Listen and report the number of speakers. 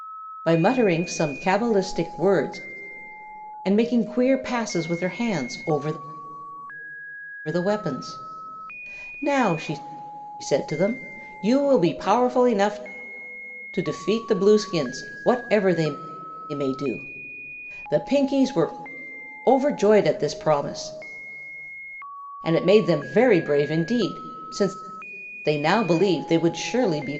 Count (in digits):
1